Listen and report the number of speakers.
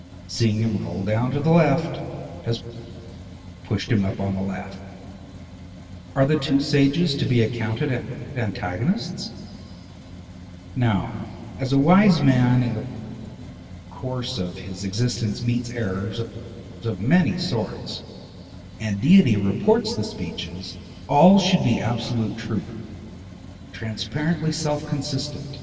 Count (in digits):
1